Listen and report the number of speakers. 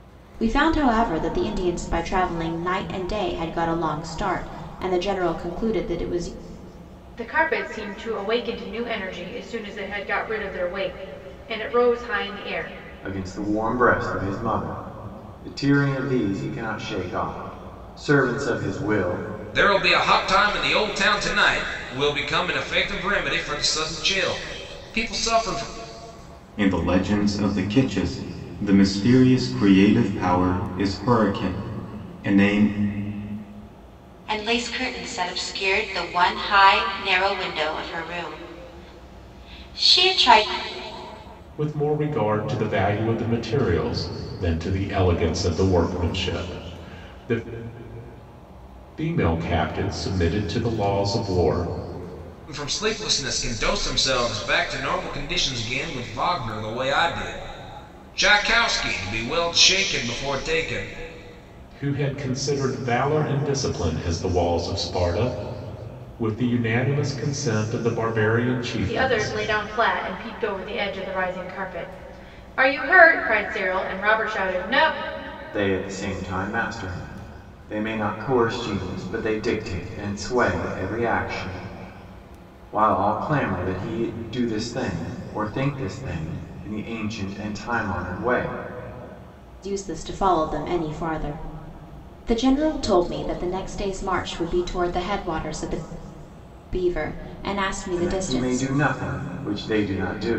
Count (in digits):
7